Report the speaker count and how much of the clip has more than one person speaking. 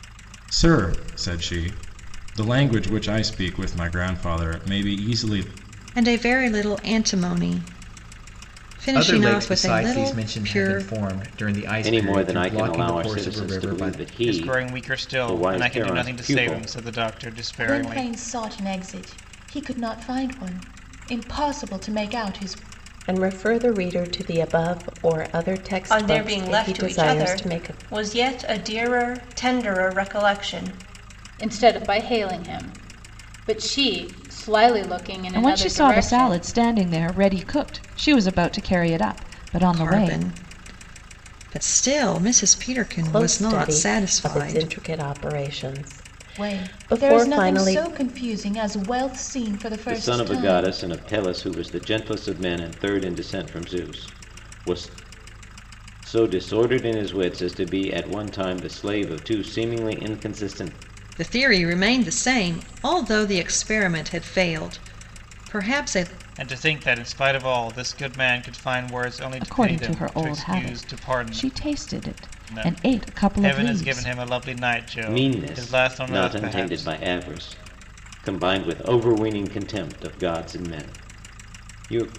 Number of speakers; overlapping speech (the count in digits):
10, about 25%